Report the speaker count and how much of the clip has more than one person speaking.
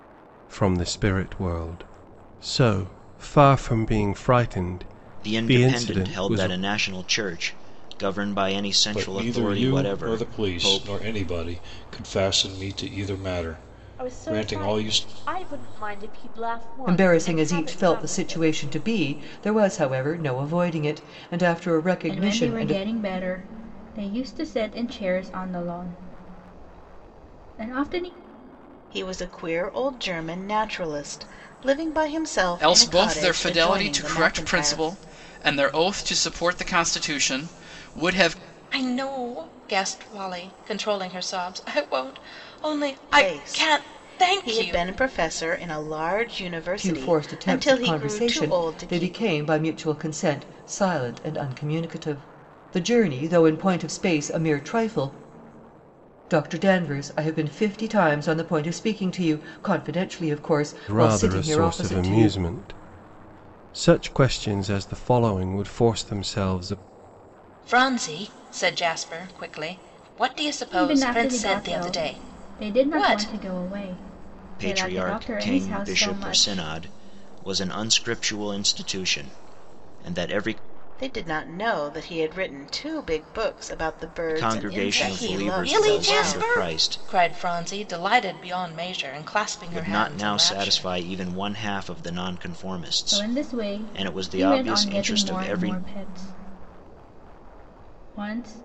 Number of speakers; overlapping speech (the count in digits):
9, about 27%